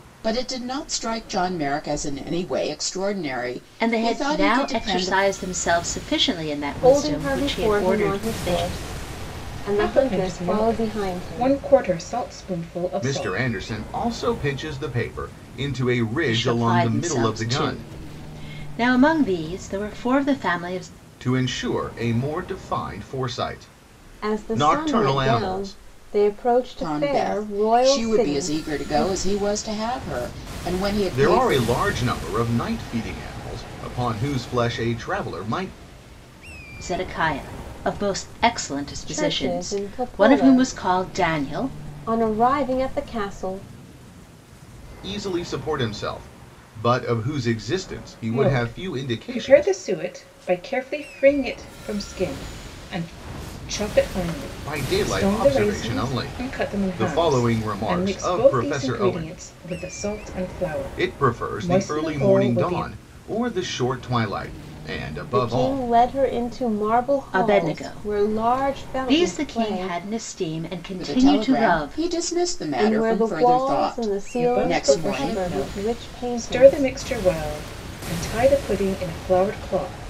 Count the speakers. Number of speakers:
five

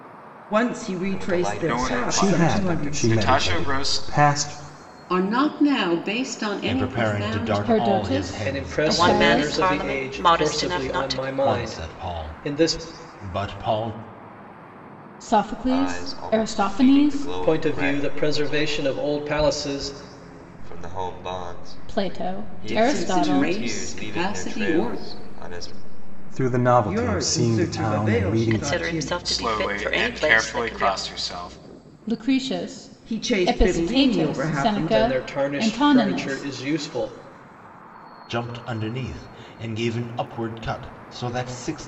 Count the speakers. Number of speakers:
nine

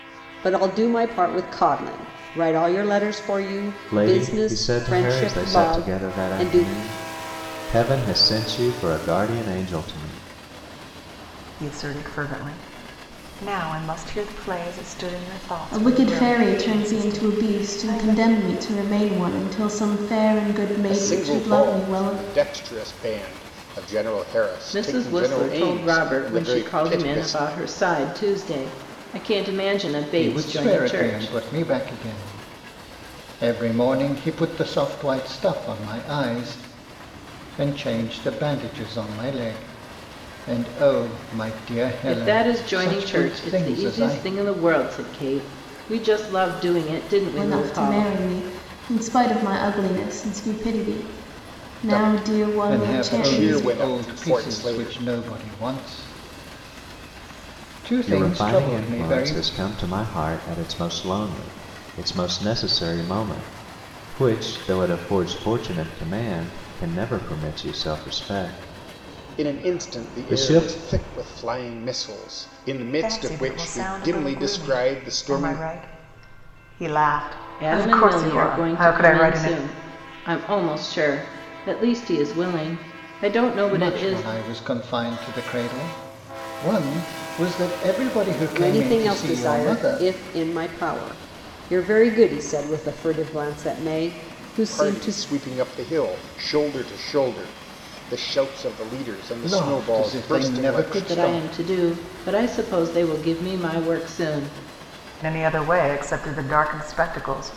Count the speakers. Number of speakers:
seven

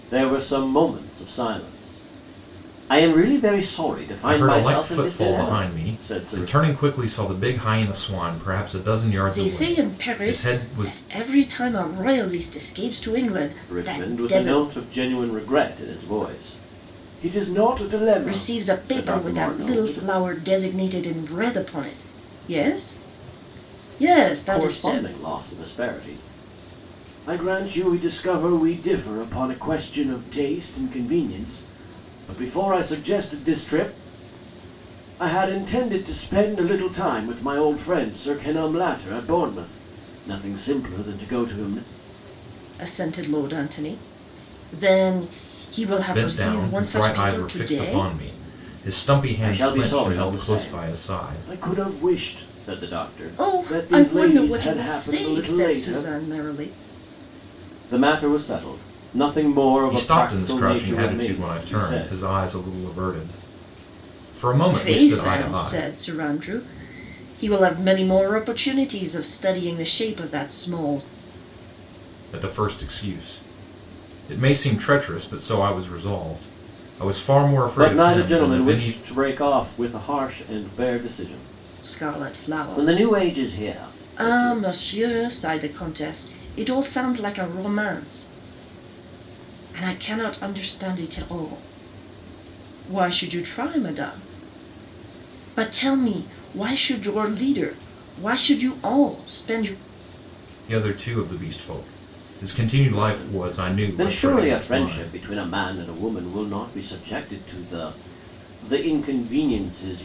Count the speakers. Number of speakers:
three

